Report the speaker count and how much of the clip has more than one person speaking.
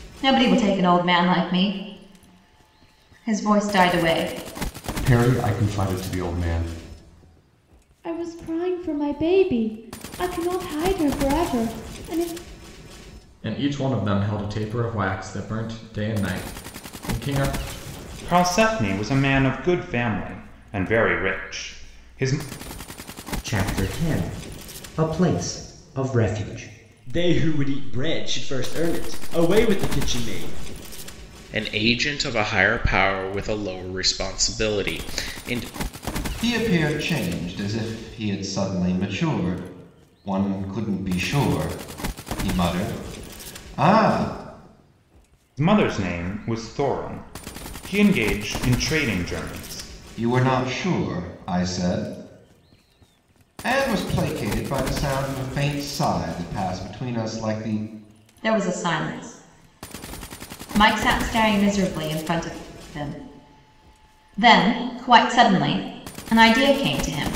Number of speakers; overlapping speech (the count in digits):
9, no overlap